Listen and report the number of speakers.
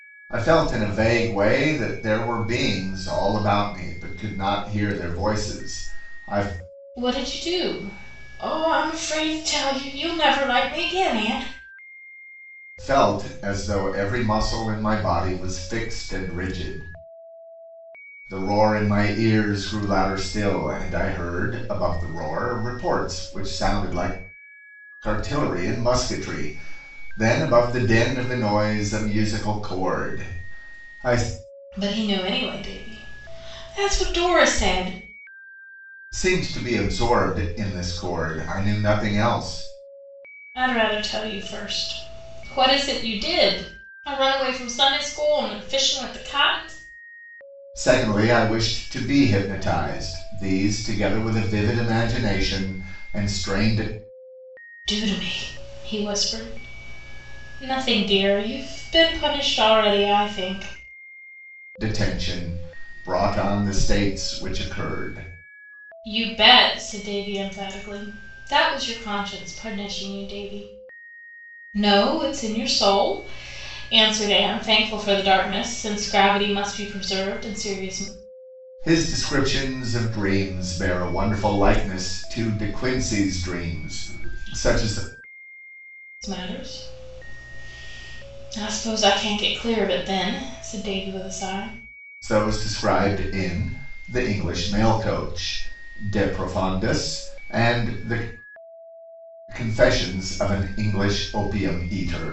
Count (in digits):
2